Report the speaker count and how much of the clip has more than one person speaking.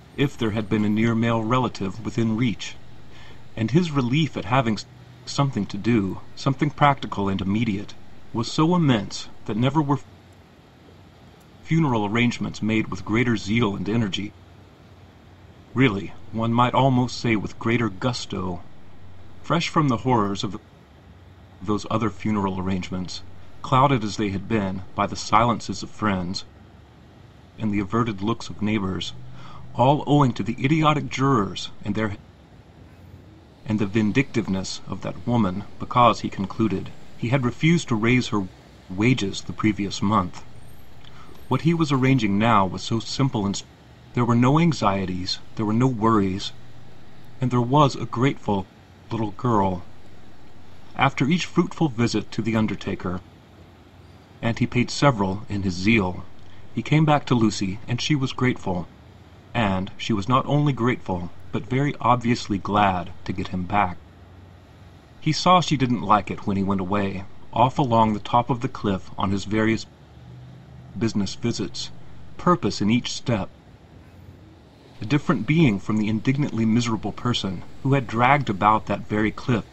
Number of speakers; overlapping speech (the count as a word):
one, no overlap